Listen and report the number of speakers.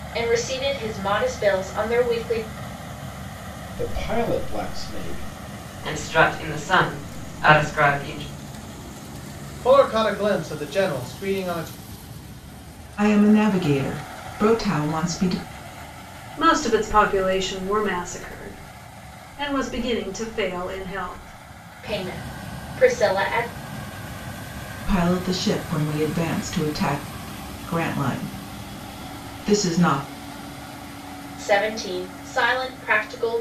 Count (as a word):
six